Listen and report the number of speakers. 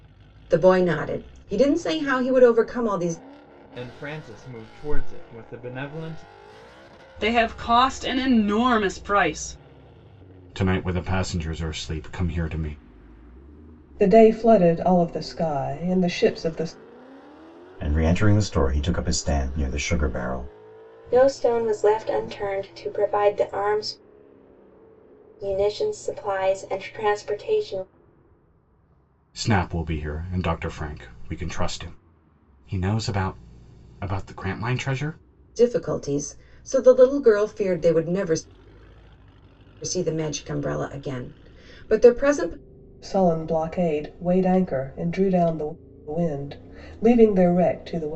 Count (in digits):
7